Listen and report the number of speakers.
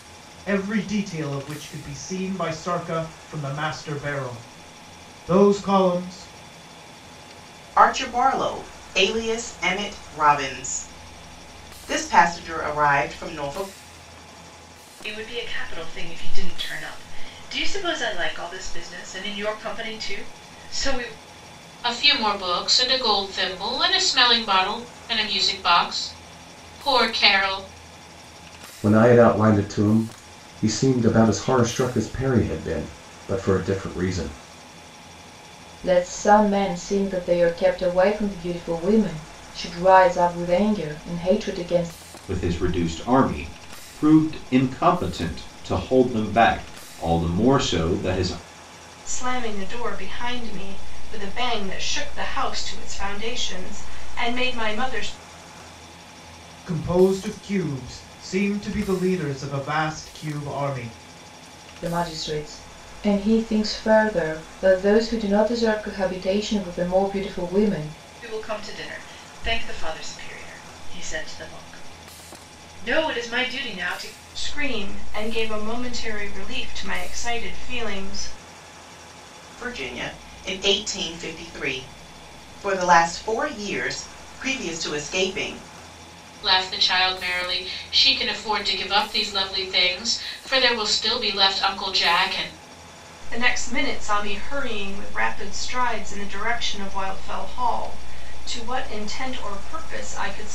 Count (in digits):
8